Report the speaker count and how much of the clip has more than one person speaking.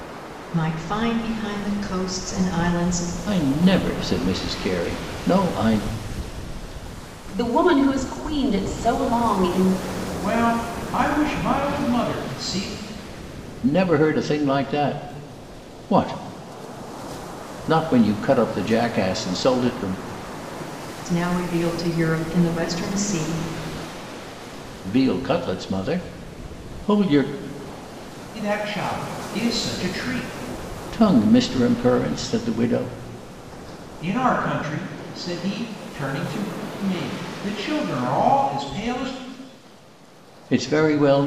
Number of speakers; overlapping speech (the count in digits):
4, no overlap